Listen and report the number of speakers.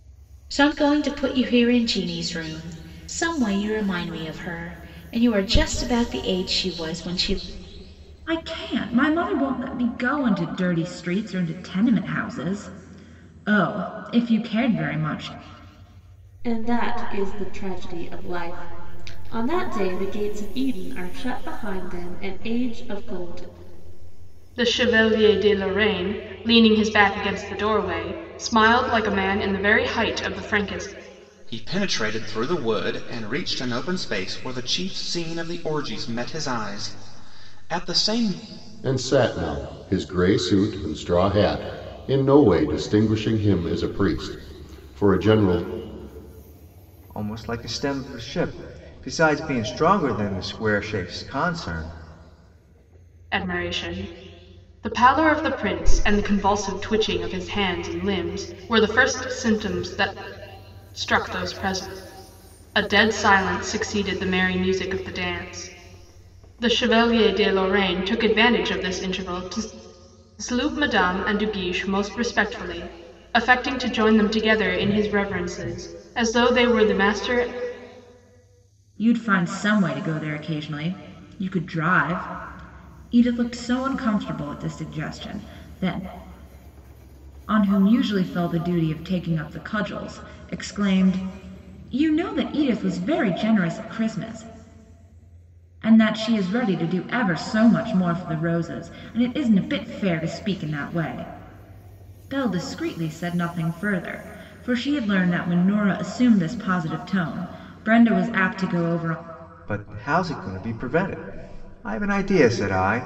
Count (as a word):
seven